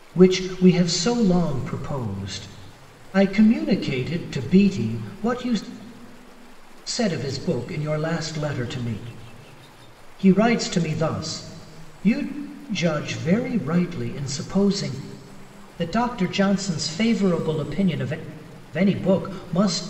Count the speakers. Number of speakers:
one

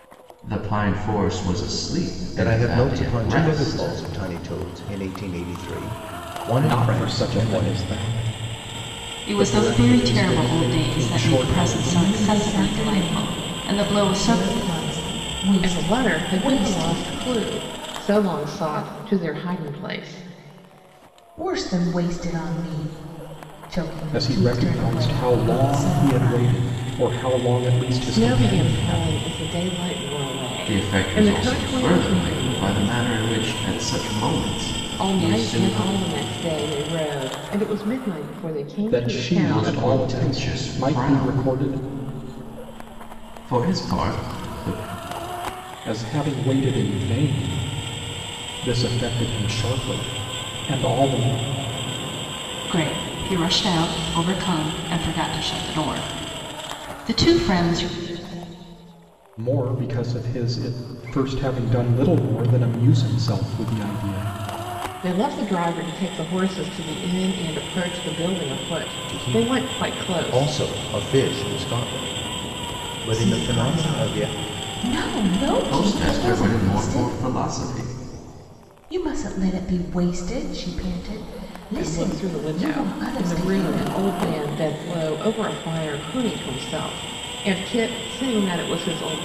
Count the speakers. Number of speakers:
six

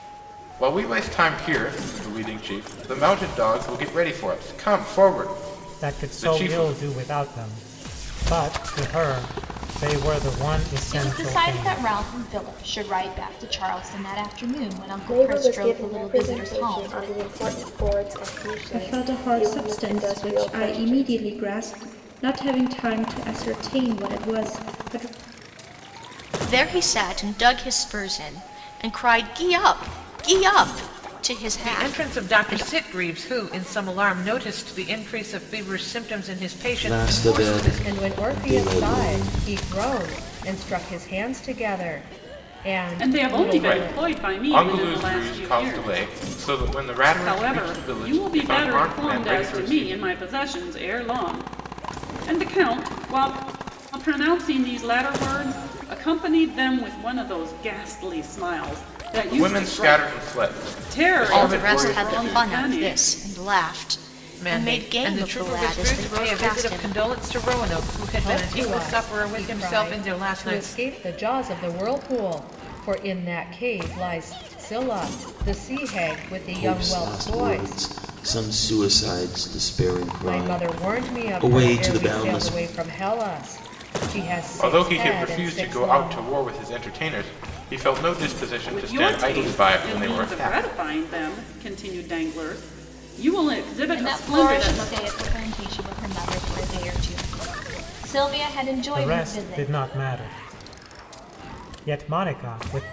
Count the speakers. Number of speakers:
ten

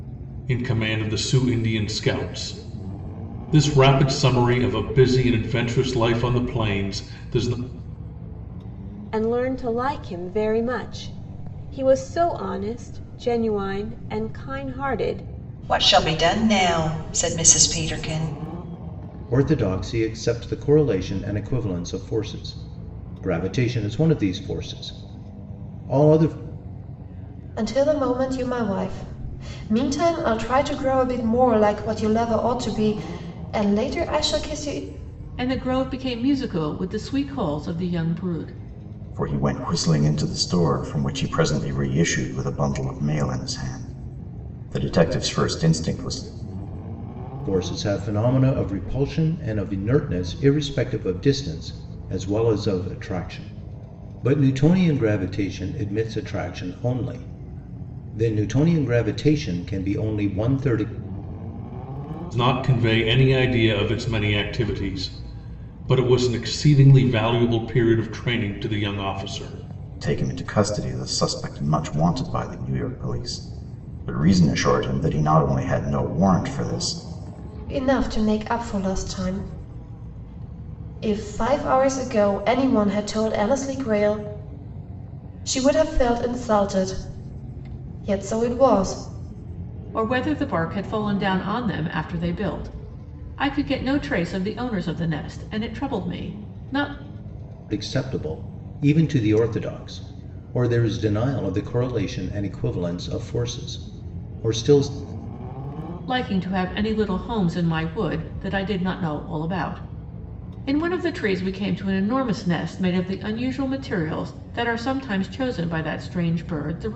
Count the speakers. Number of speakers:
seven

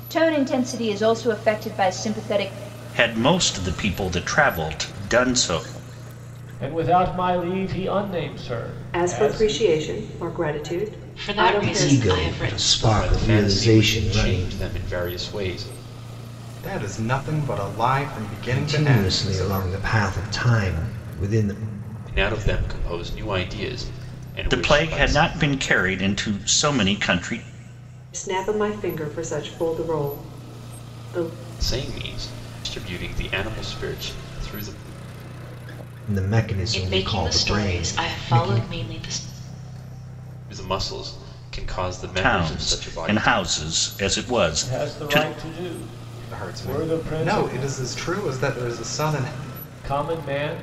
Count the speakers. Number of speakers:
eight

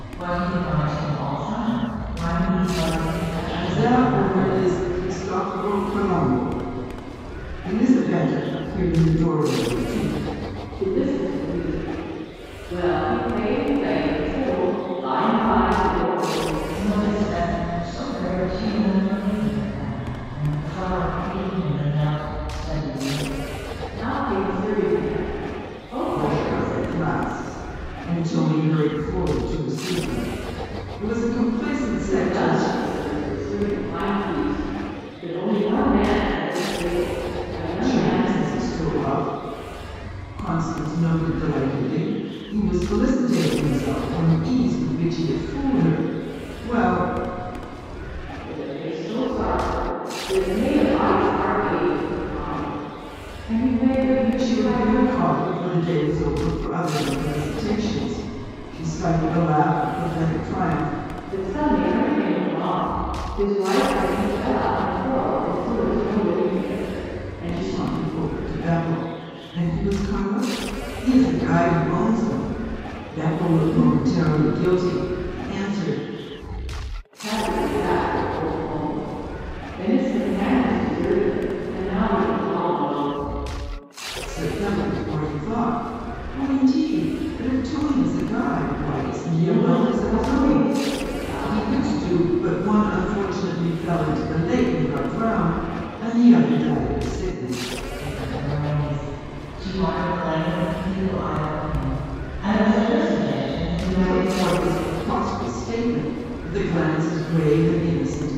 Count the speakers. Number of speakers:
three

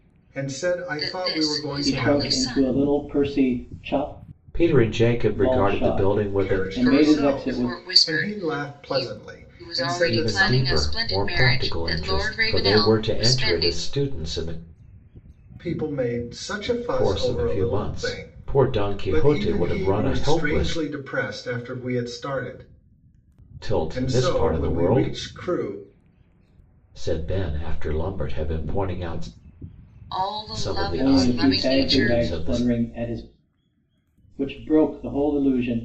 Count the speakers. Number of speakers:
four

